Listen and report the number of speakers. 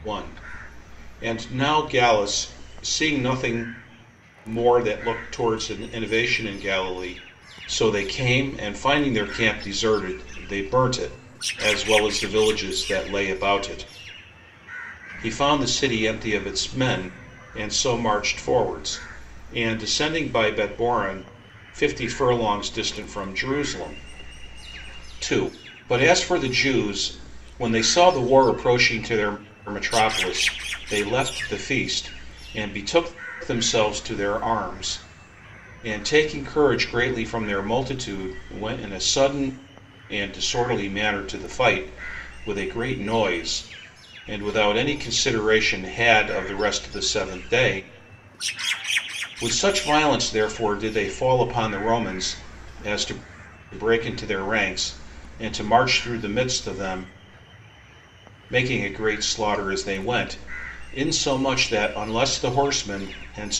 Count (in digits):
1